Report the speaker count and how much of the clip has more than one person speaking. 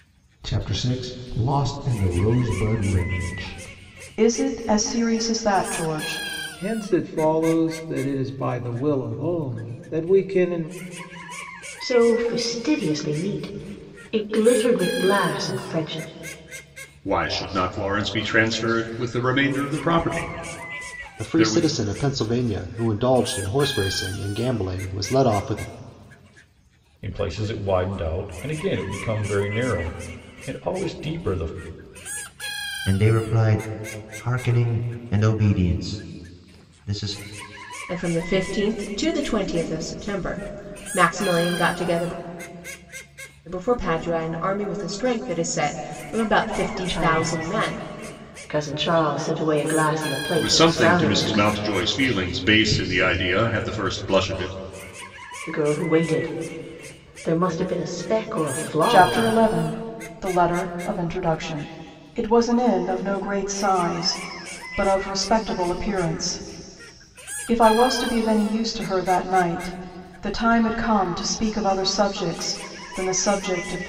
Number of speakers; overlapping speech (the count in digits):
9, about 4%